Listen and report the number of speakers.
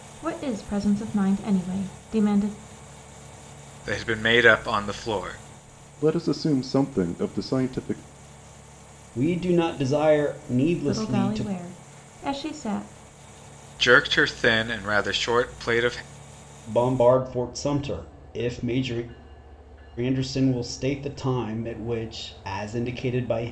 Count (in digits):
4